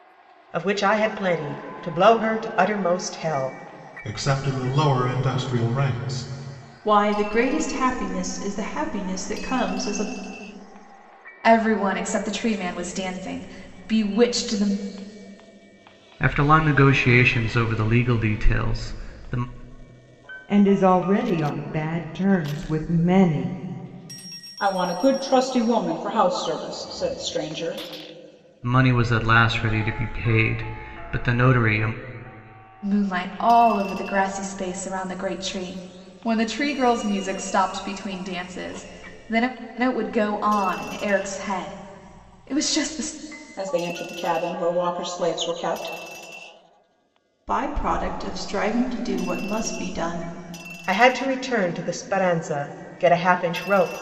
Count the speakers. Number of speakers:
seven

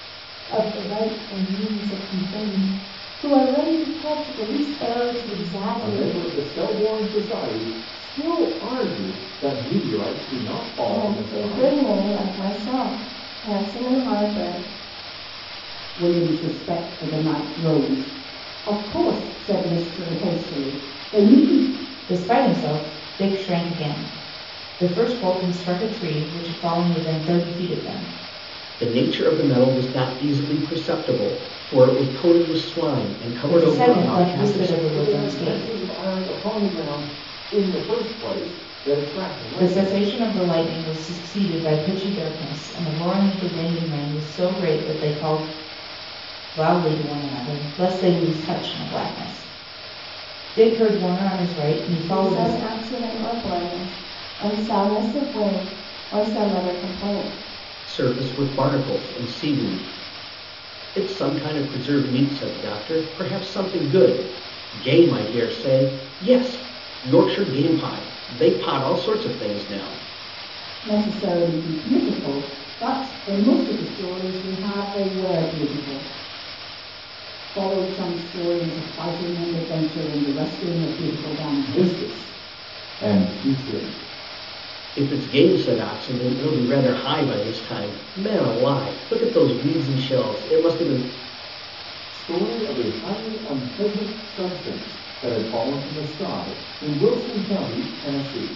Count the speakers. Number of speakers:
six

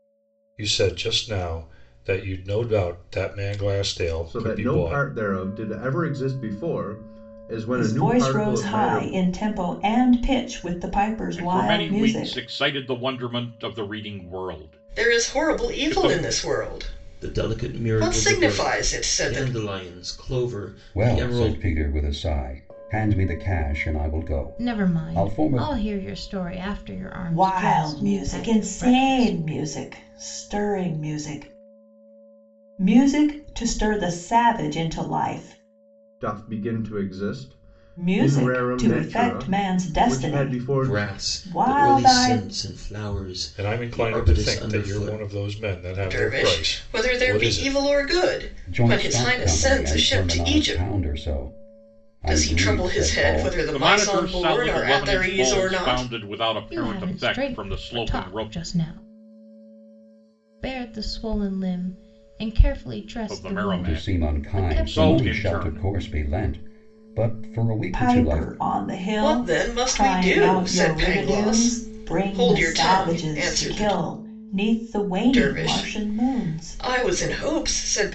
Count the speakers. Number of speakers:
eight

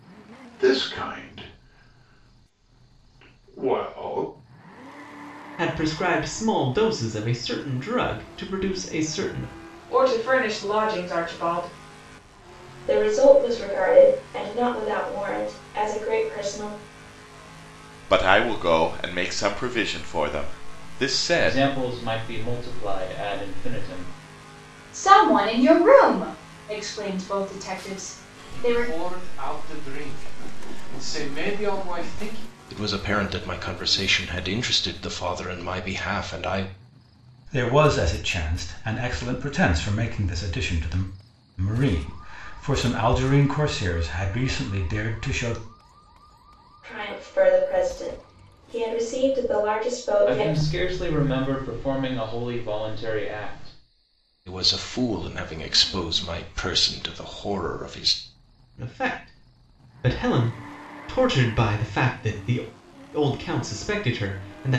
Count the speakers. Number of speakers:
ten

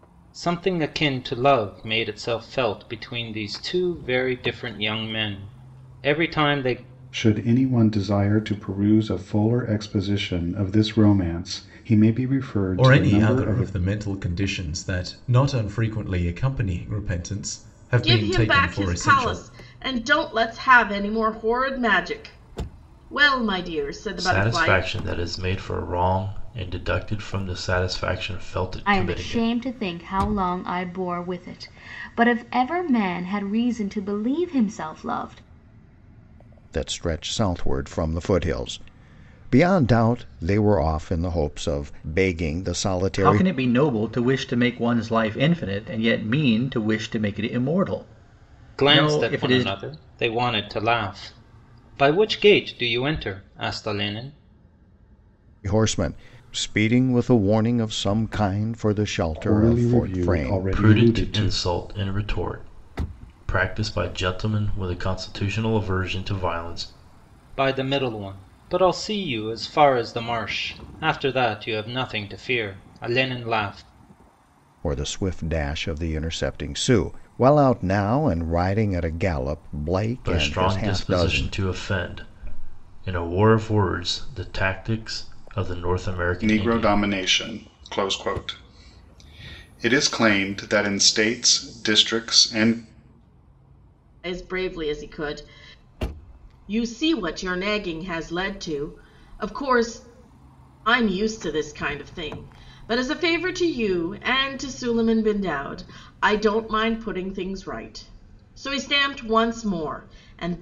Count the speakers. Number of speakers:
eight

